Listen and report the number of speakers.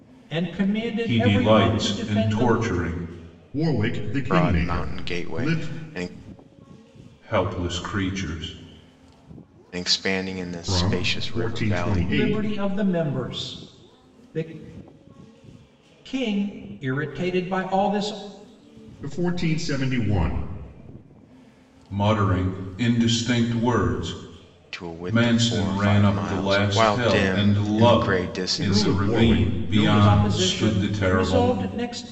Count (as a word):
four